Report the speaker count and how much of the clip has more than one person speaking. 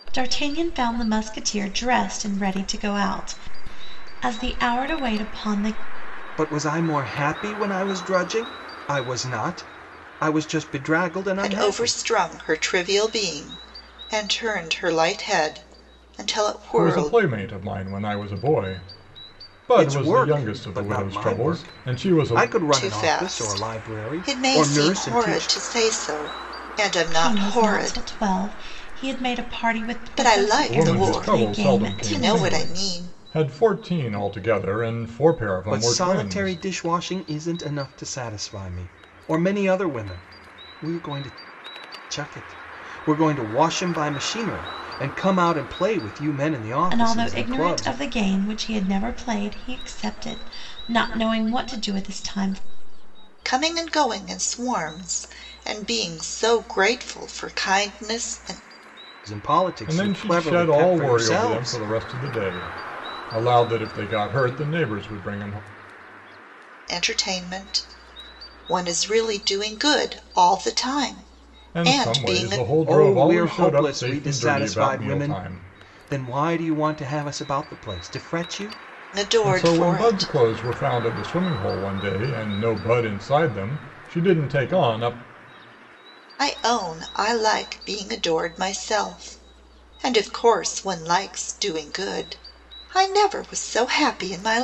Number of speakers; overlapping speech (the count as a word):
four, about 21%